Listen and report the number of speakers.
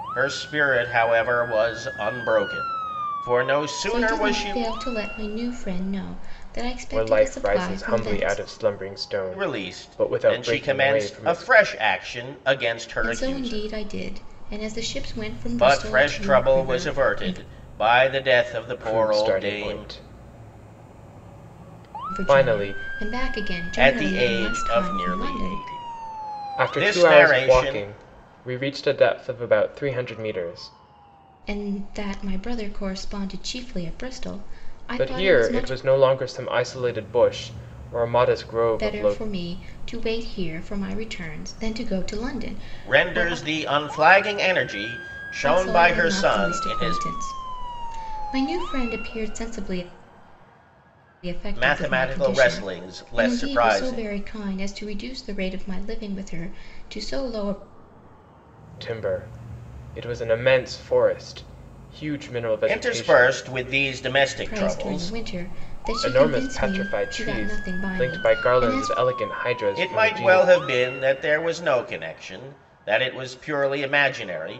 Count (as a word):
three